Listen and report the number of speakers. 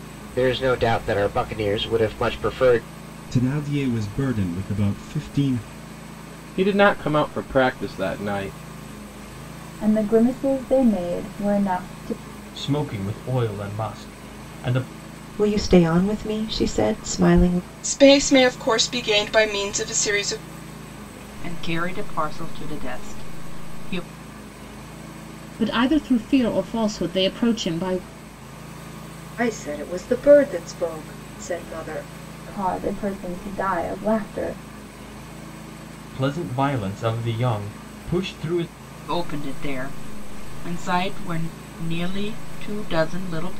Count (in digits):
10